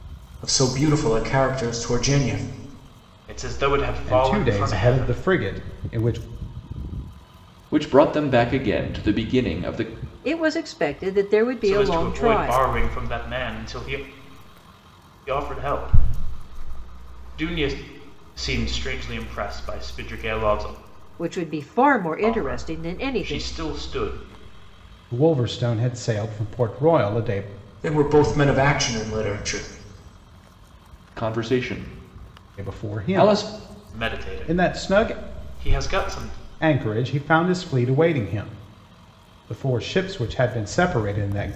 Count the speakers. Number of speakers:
five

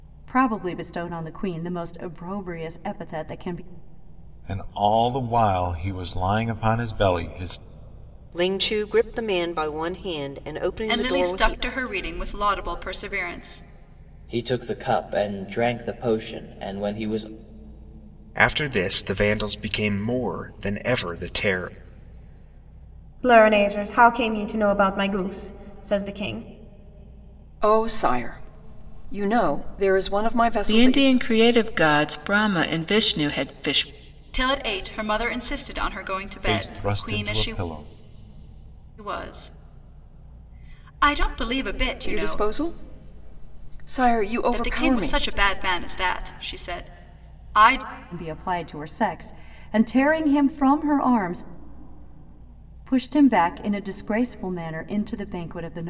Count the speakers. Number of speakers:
nine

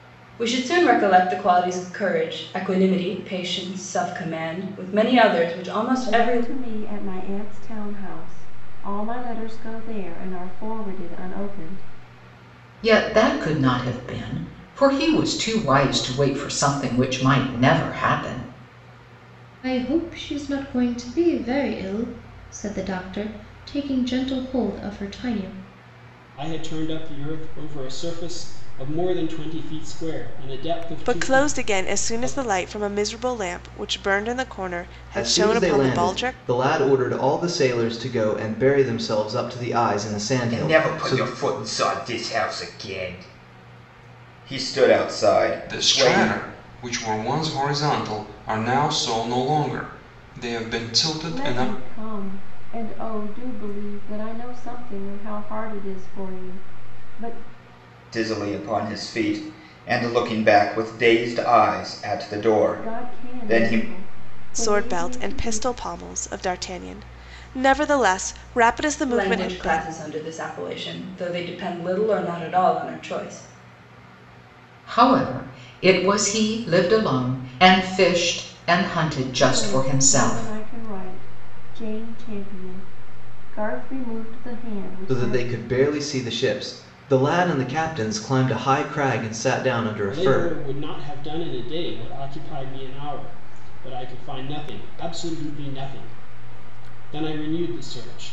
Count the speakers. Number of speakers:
nine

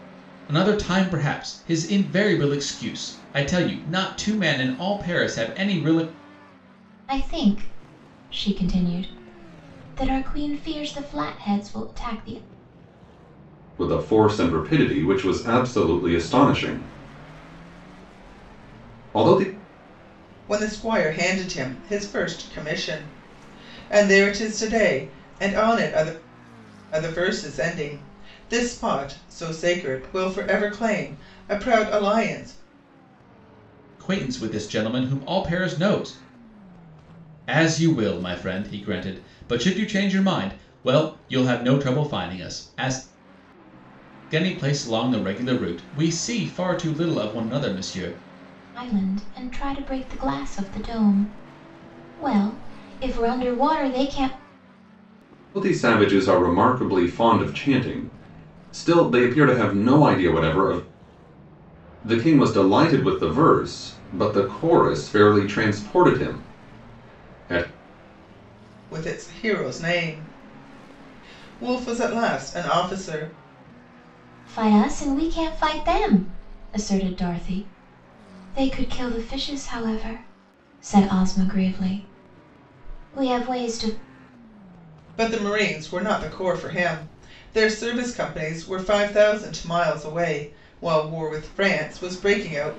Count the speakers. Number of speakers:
four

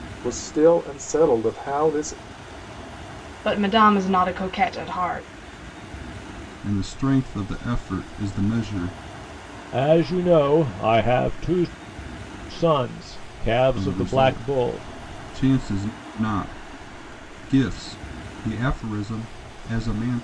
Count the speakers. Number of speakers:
four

